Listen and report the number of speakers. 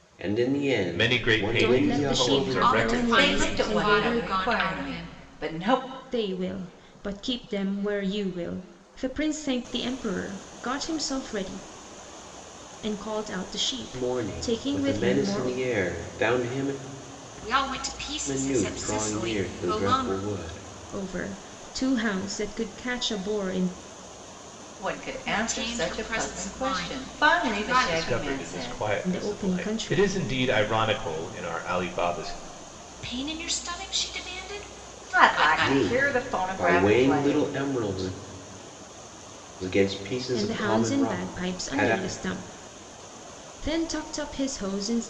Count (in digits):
5